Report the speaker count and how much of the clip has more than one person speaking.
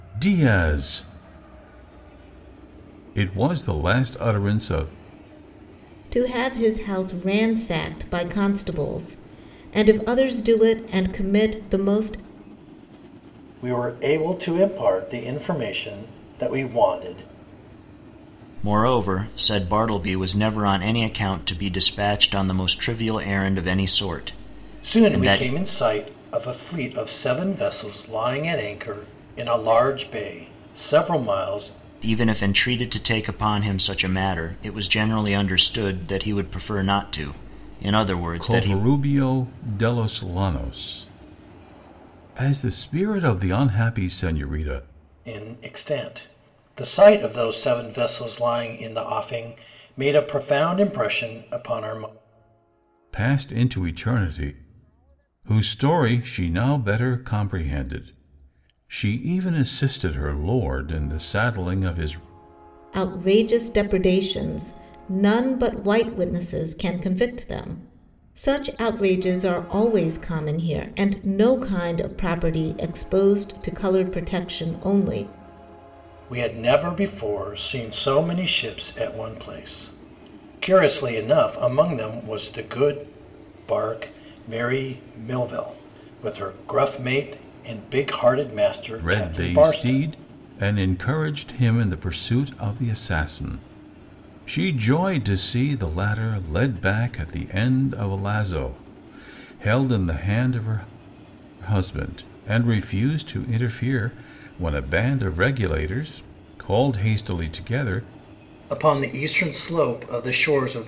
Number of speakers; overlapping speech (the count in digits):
4, about 2%